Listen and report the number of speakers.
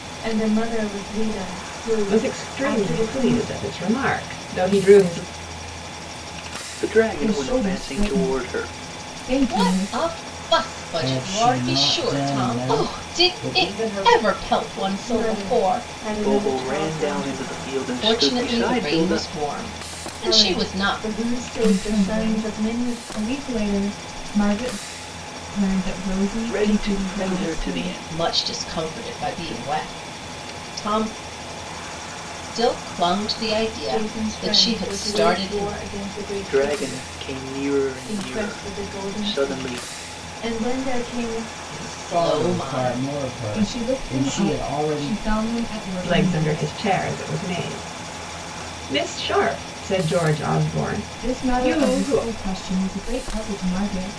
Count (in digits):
6